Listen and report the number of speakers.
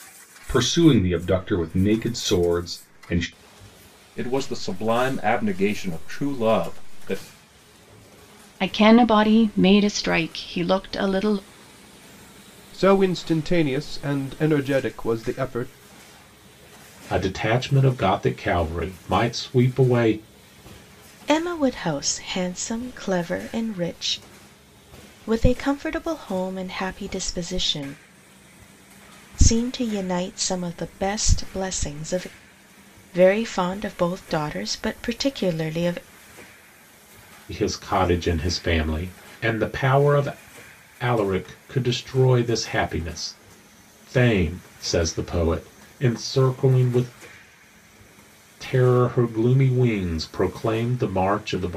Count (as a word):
six